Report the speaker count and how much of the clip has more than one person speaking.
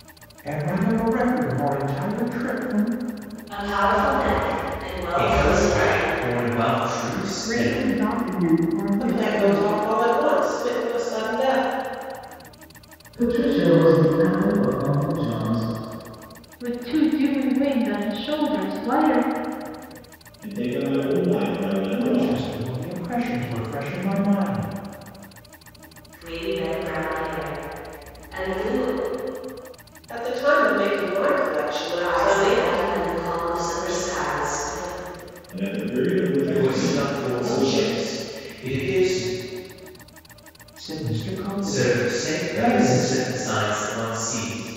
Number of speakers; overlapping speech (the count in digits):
8, about 16%